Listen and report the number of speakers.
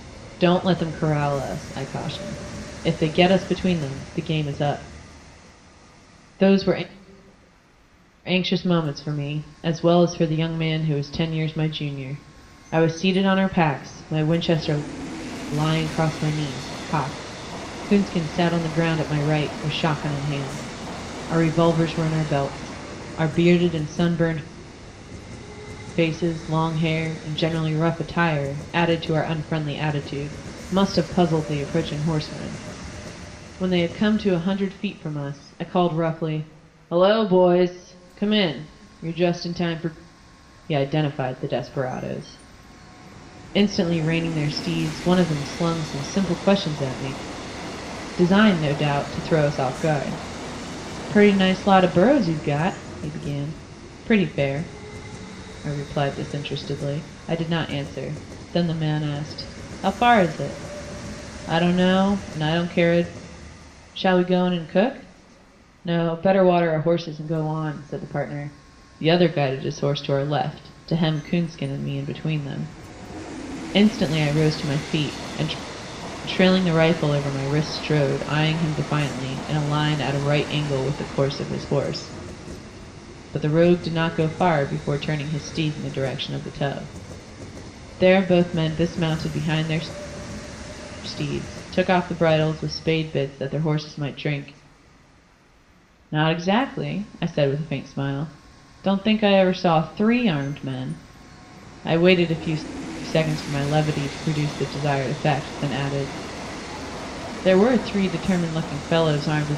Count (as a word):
one